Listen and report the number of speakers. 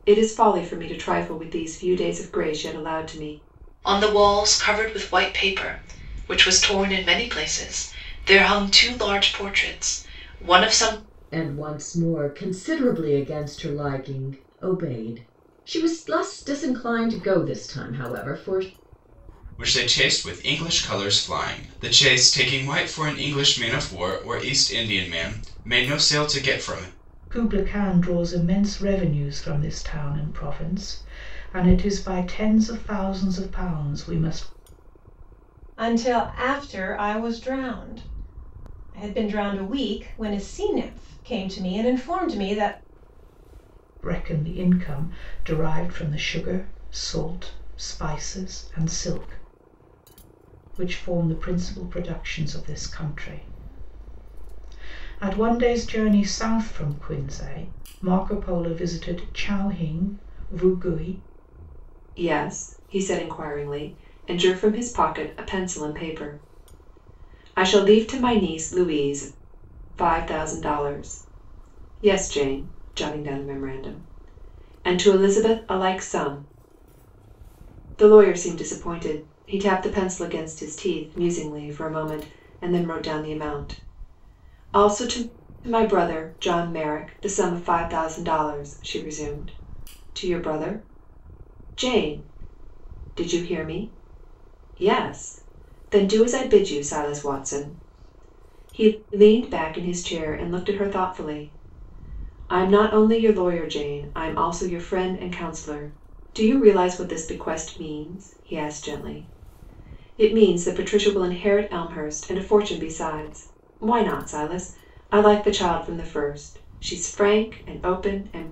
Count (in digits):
6